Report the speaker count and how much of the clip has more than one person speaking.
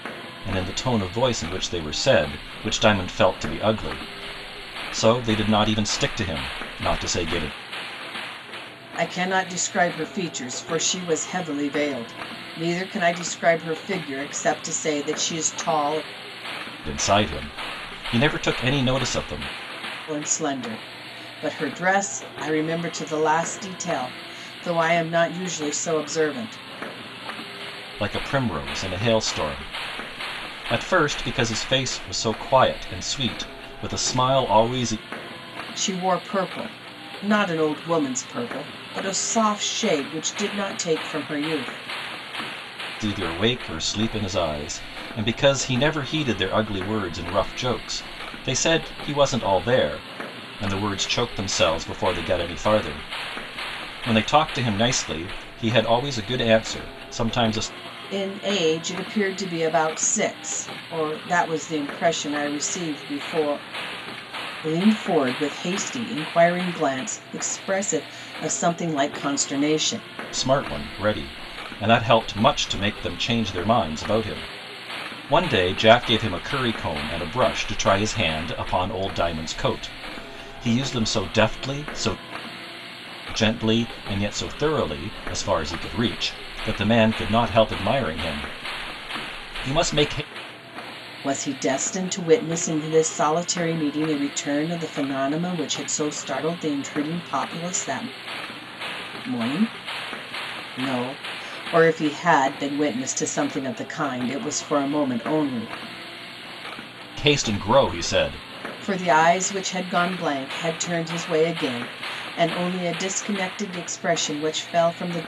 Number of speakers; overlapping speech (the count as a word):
two, no overlap